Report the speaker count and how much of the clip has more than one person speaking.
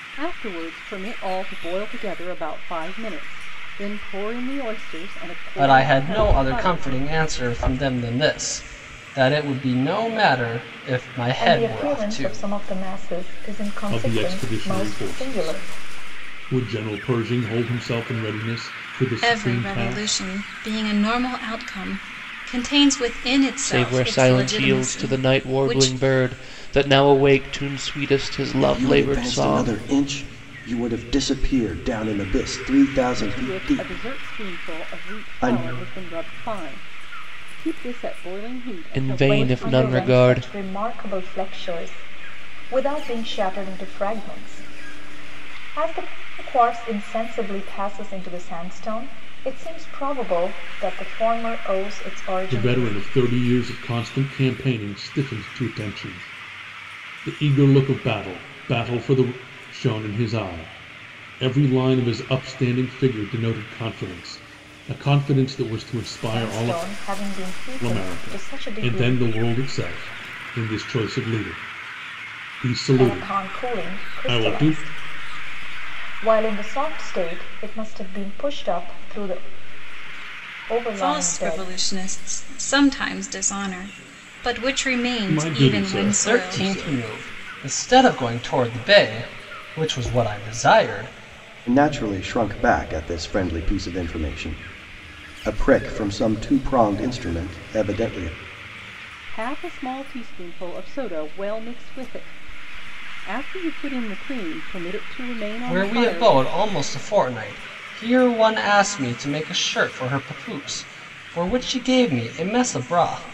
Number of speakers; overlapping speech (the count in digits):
7, about 18%